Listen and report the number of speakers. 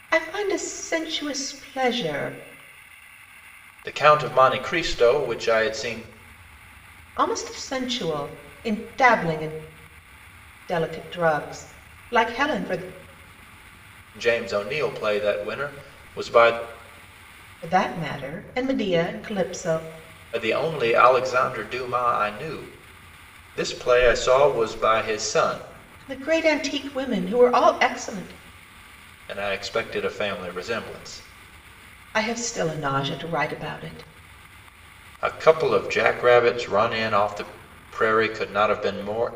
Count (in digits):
2